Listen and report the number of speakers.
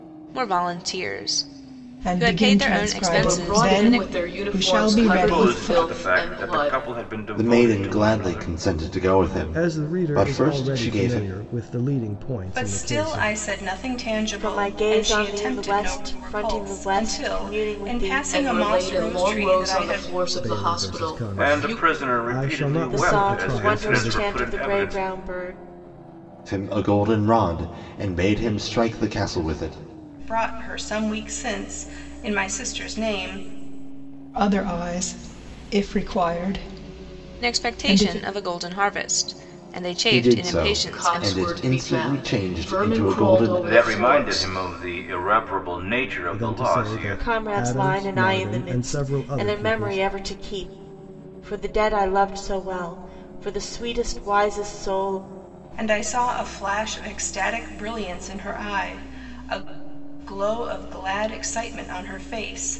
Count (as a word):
eight